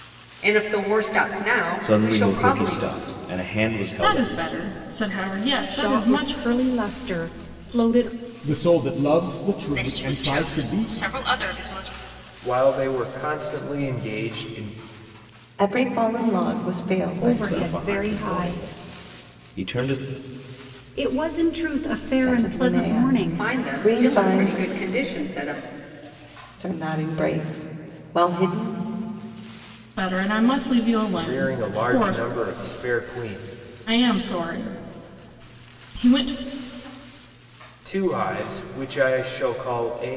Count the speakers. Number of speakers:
eight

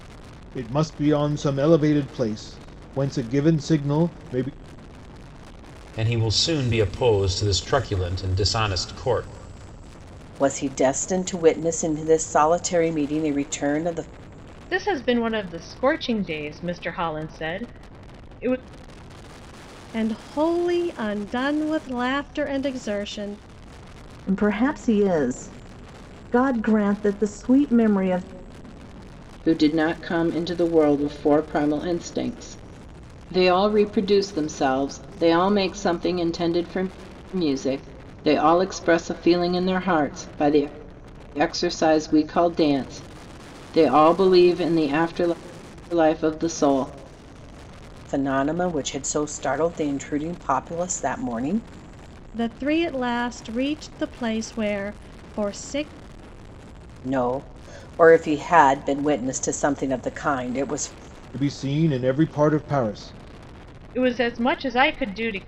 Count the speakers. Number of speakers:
seven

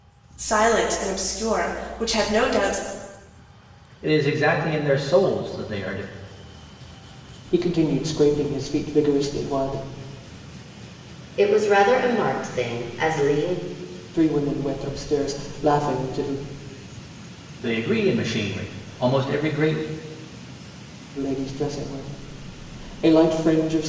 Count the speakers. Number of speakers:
four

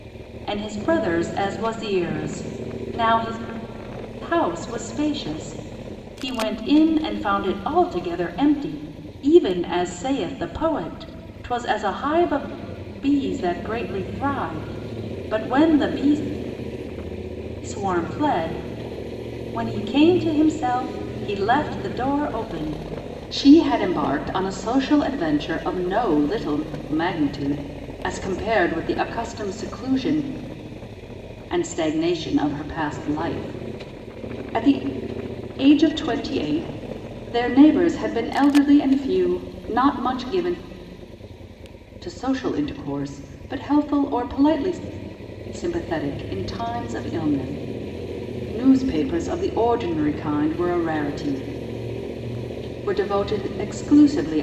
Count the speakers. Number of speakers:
one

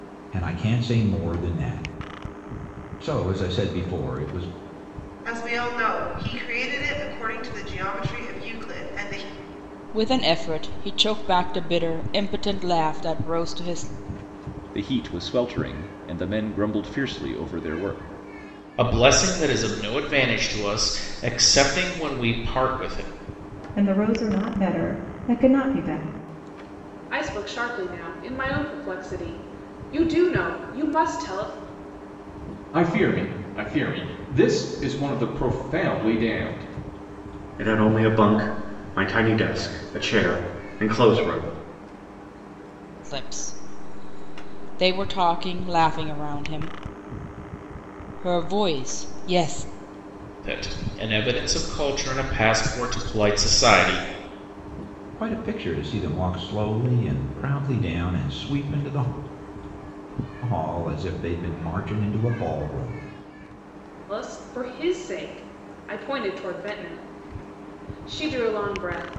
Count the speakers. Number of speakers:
nine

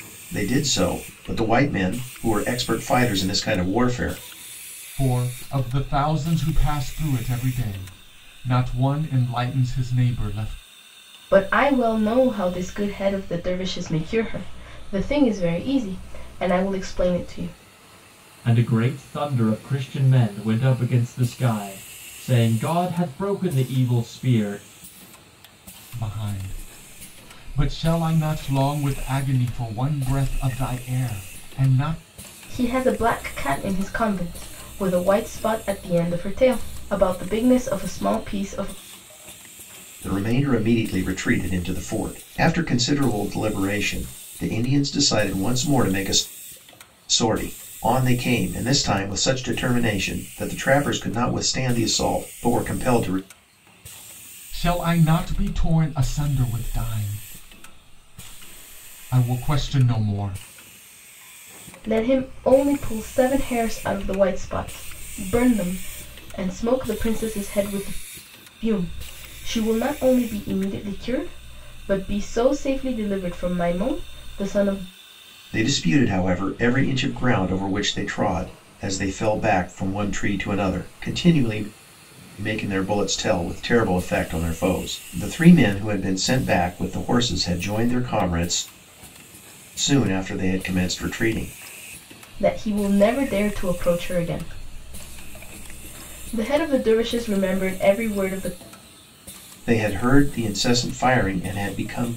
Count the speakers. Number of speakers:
four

